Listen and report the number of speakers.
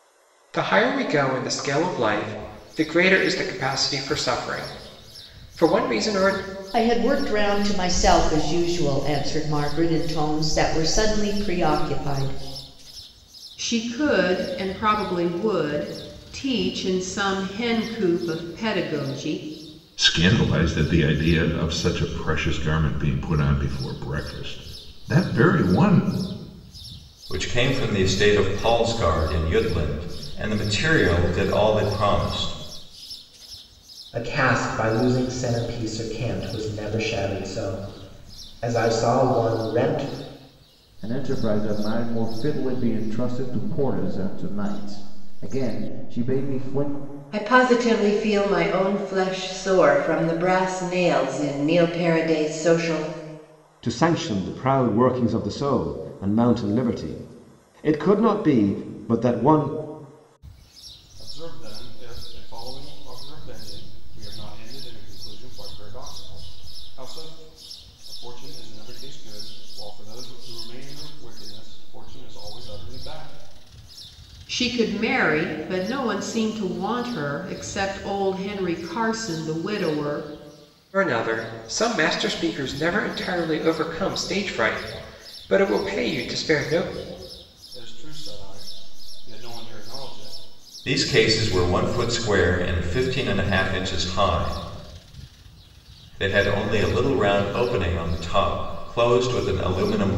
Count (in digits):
10